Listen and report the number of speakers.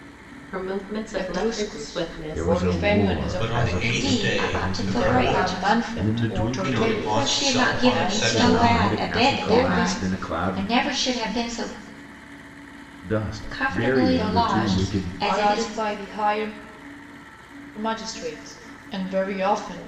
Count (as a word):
five